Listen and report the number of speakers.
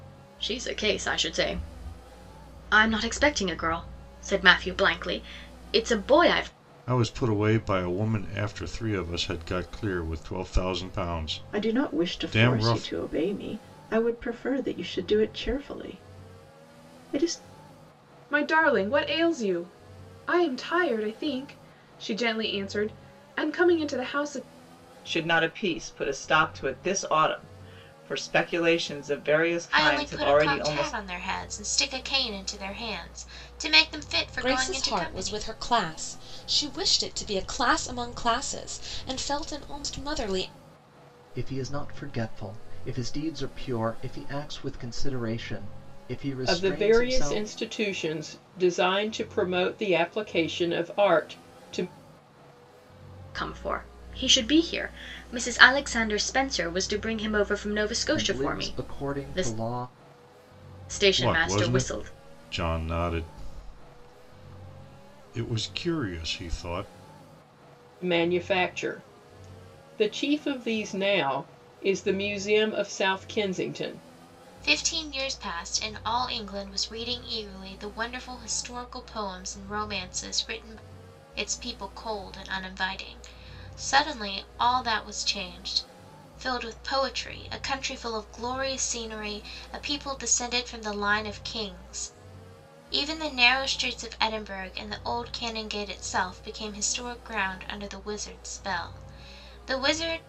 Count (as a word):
nine